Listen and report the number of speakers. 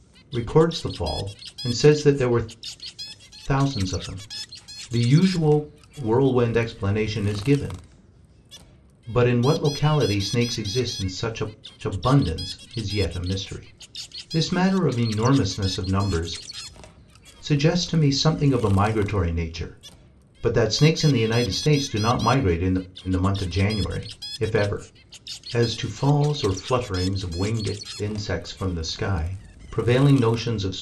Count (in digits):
1